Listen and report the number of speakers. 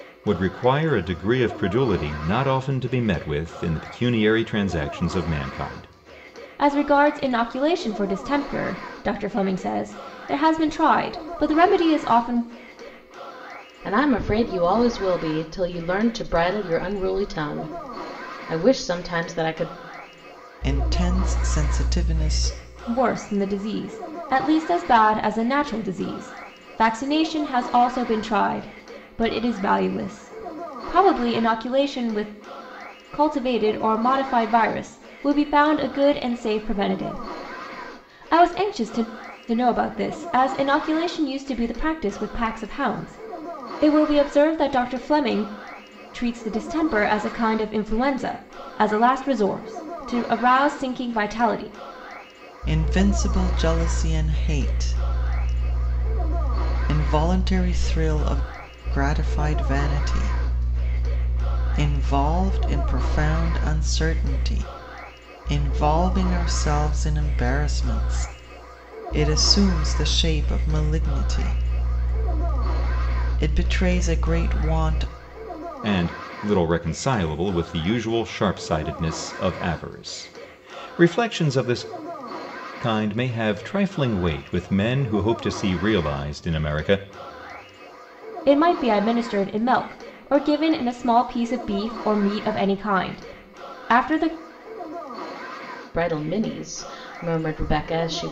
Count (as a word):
four